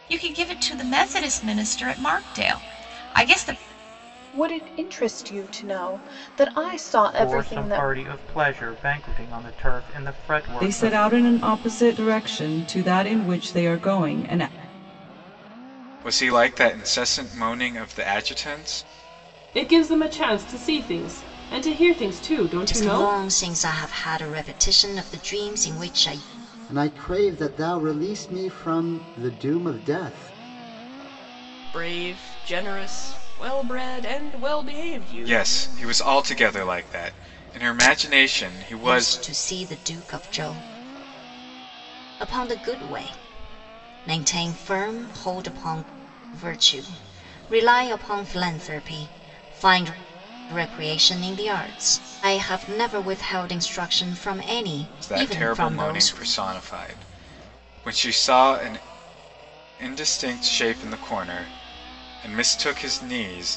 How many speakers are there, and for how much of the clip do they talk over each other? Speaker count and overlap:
nine, about 6%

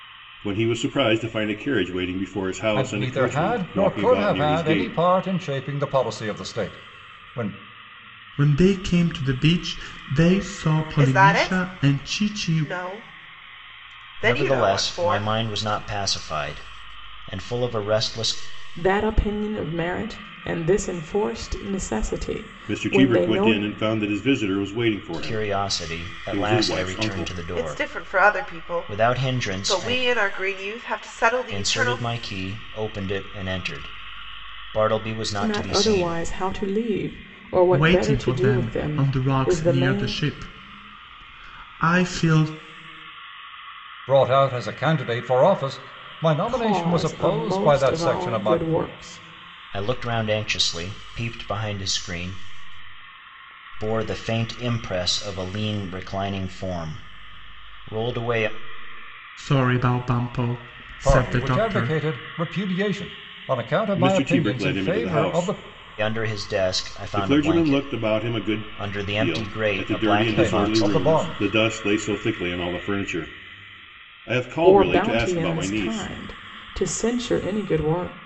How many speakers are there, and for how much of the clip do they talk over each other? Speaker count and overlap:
six, about 34%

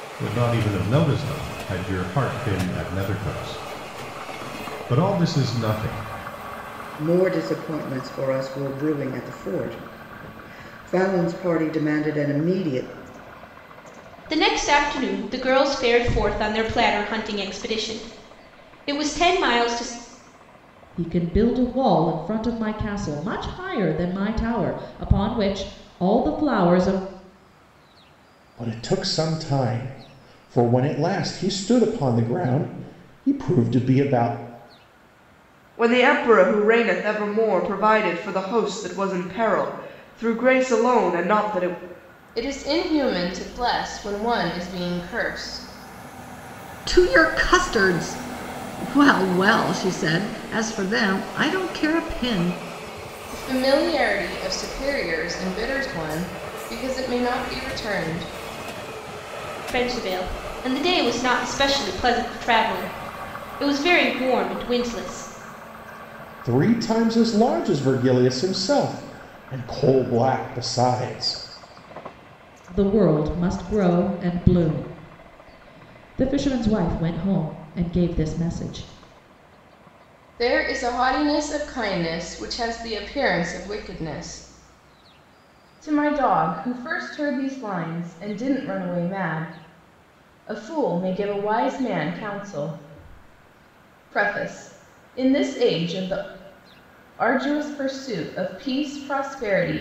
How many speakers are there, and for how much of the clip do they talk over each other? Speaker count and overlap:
eight, no overlap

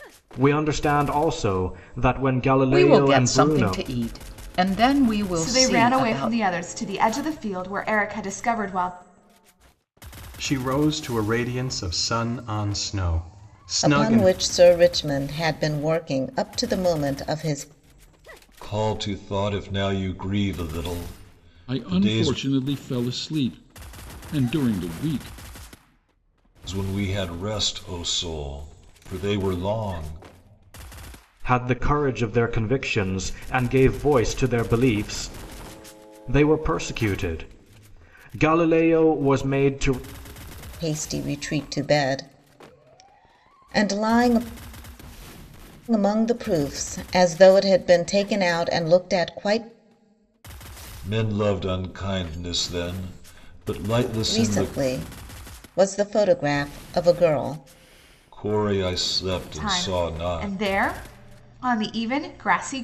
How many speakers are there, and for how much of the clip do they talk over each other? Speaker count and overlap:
seven, about 8%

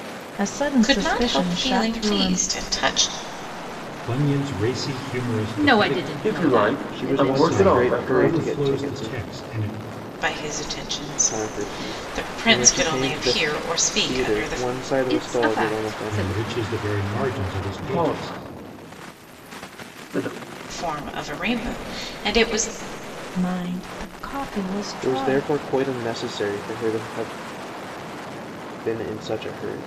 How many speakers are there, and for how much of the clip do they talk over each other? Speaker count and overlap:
six, about 37%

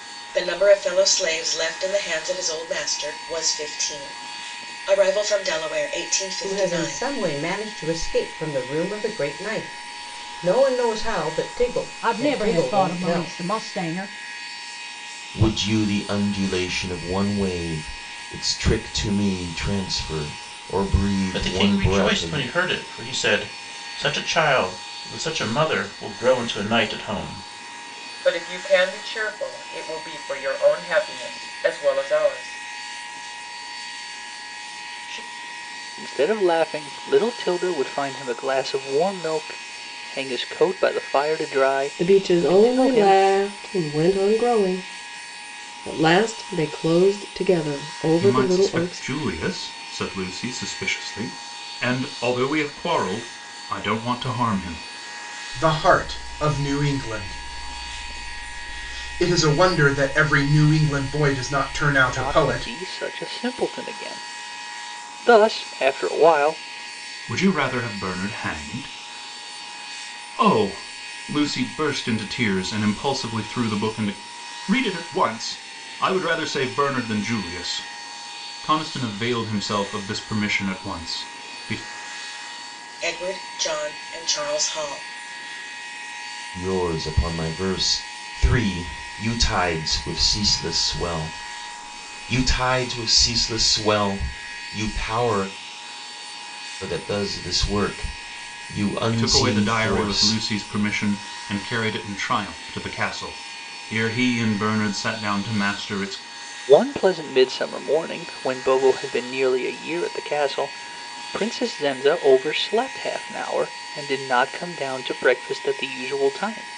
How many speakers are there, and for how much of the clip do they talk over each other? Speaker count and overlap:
ten, about 6%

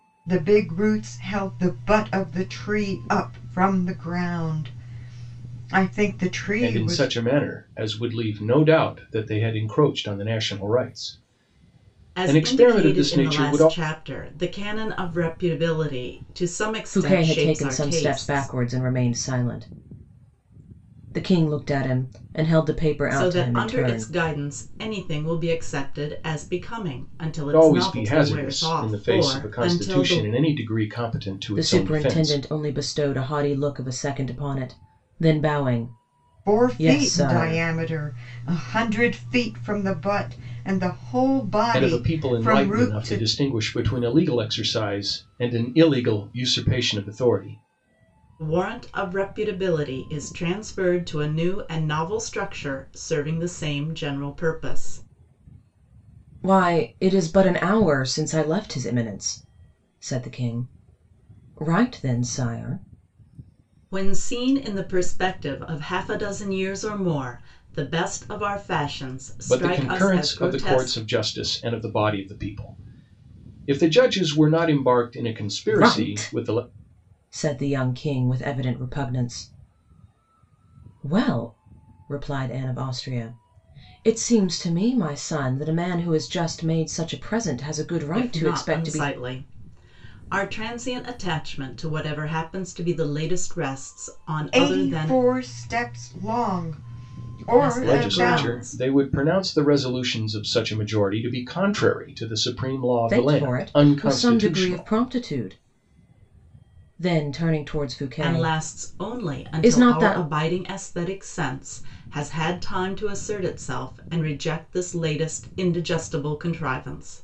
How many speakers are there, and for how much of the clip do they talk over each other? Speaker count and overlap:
four, about 18%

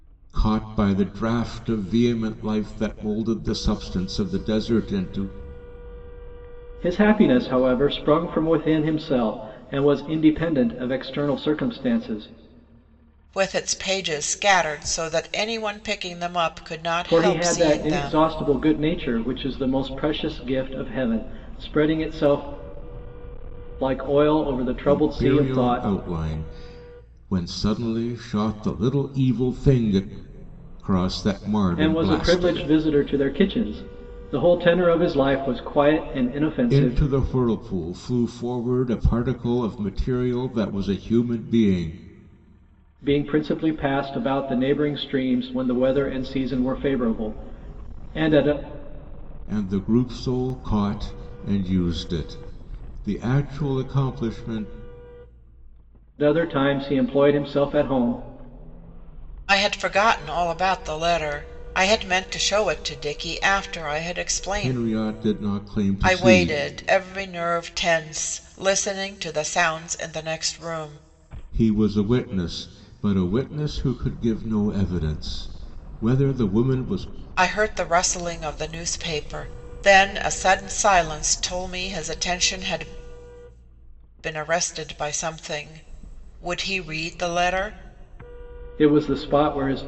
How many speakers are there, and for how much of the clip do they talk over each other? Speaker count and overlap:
three, about 5%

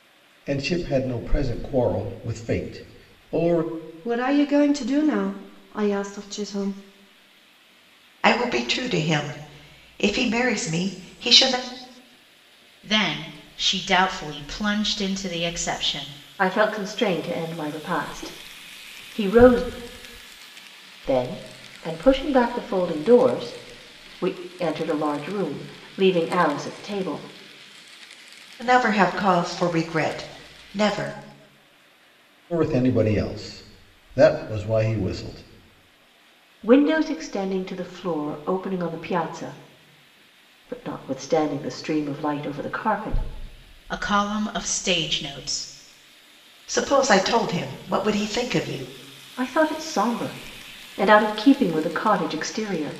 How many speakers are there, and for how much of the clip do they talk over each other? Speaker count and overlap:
five, no overlap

